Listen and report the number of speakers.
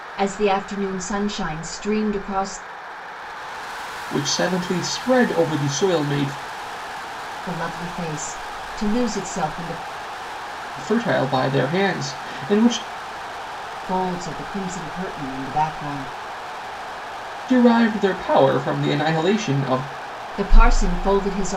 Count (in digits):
2